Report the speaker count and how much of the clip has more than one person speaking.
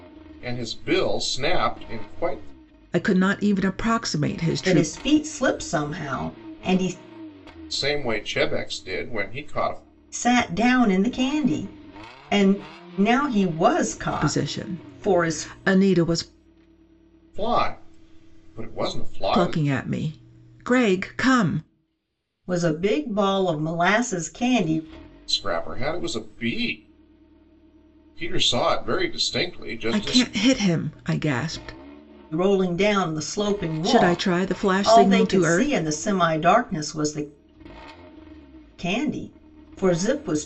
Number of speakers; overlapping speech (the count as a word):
three, about 10%